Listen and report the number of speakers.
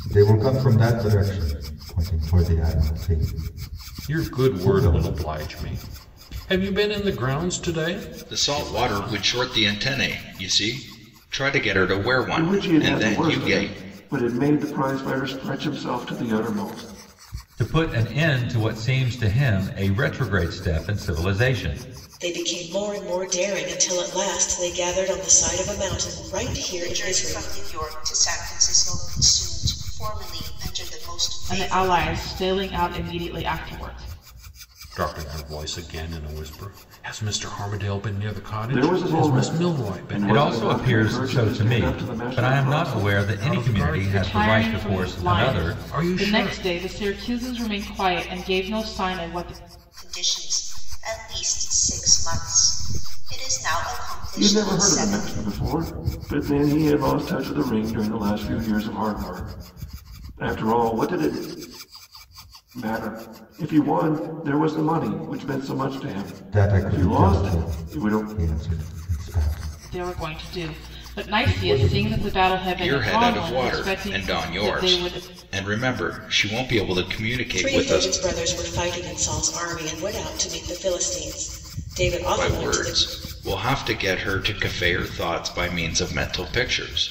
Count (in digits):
8